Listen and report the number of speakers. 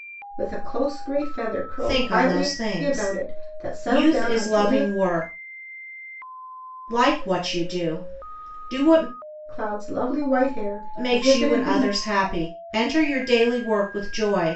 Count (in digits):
2